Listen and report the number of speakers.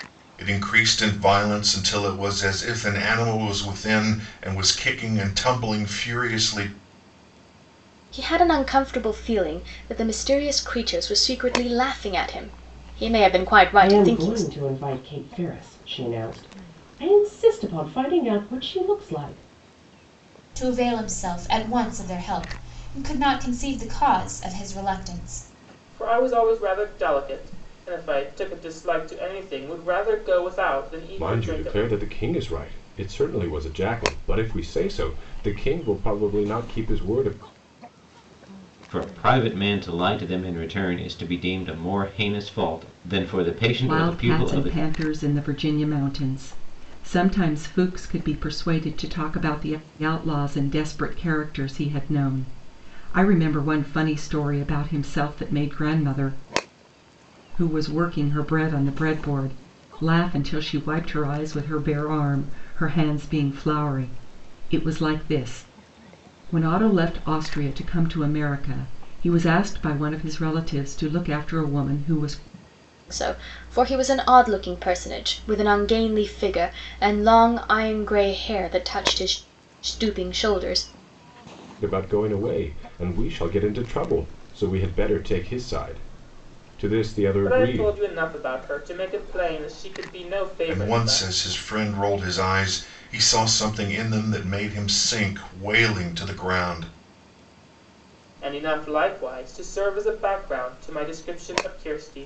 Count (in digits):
8